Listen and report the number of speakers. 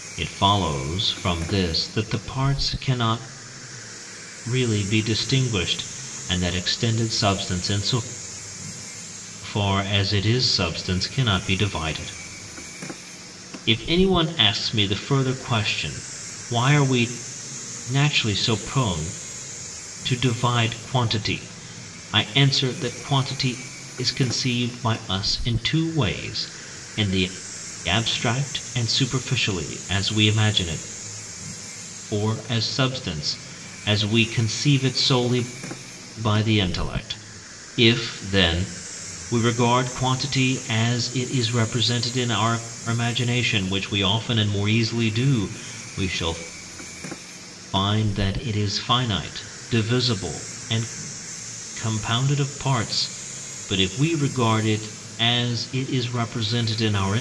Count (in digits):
1